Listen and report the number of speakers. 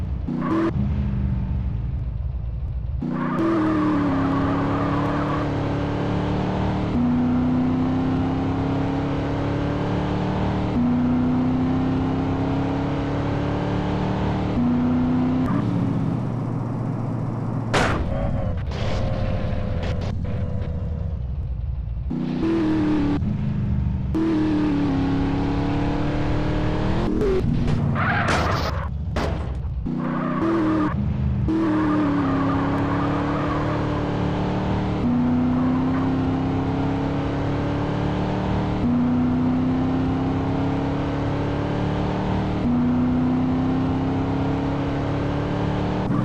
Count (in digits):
0